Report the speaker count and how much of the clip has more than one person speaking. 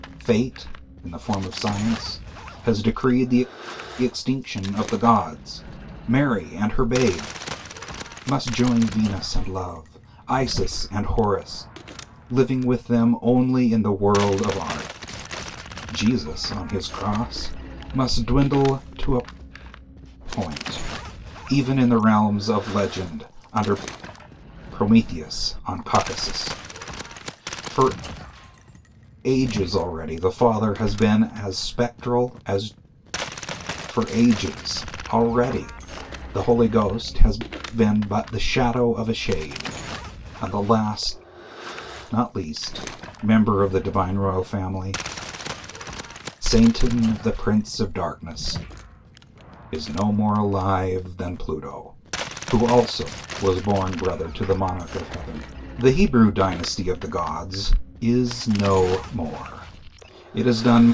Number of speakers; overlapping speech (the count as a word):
one, no overlap